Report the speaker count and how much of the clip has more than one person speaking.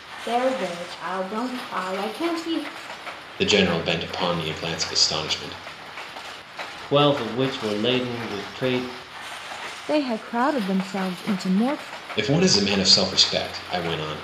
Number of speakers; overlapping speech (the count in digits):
4, no overlap